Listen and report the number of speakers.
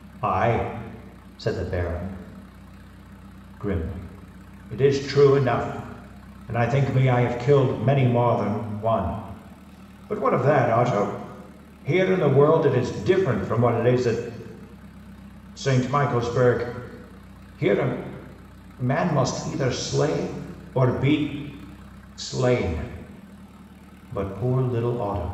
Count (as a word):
one